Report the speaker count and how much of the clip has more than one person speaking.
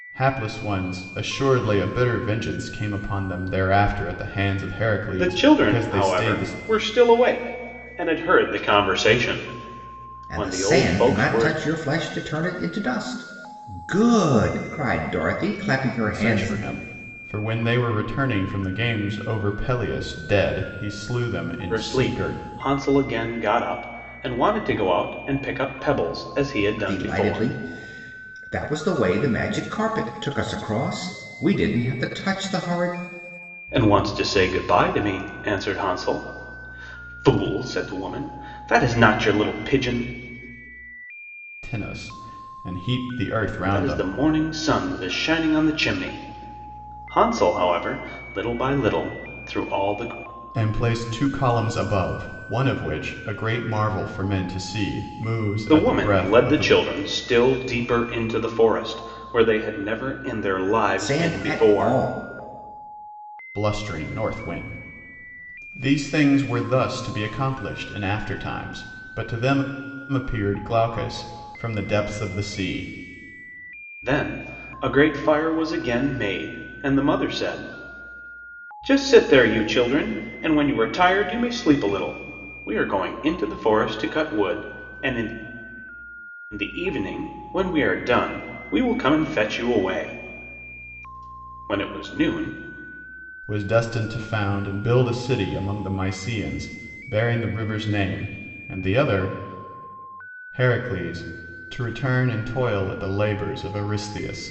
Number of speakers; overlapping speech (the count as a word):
three, about 7%